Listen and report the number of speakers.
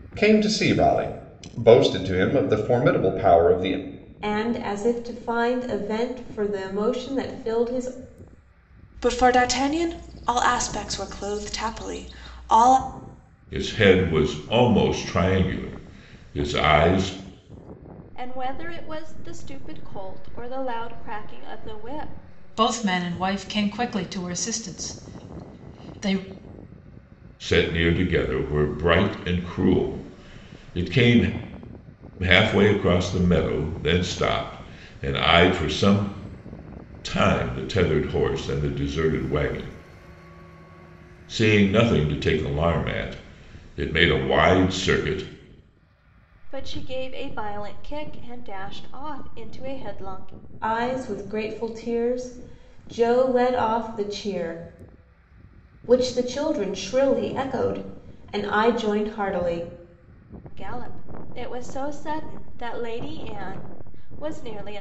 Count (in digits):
6